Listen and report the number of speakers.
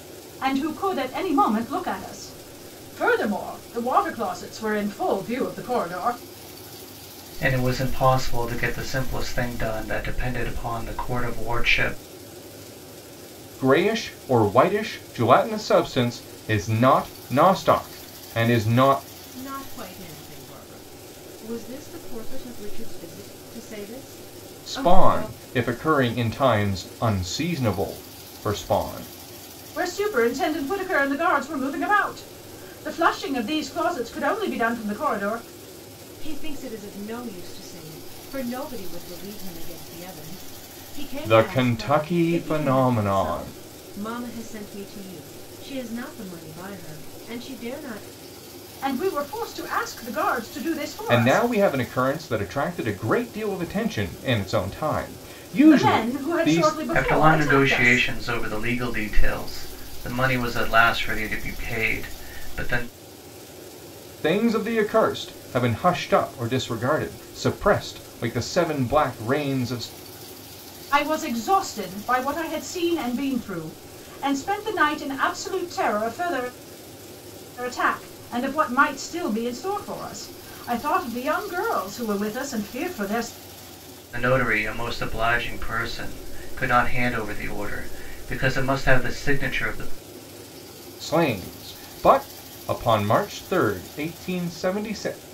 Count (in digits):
4